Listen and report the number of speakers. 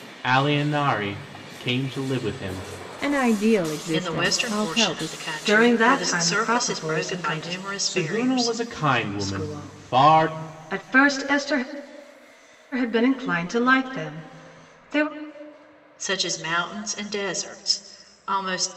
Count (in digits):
4